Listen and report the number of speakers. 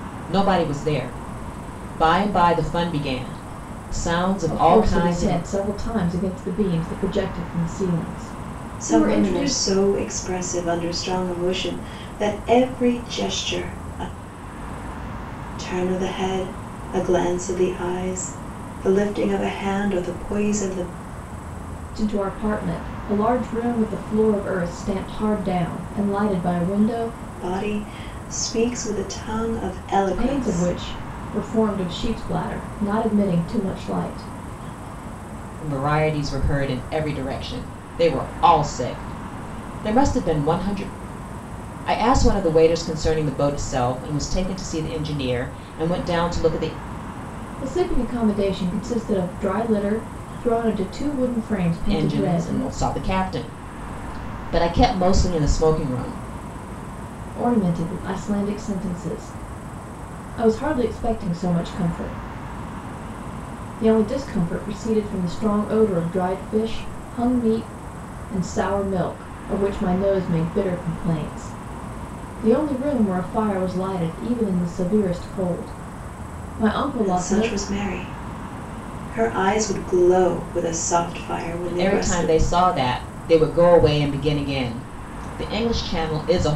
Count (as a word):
three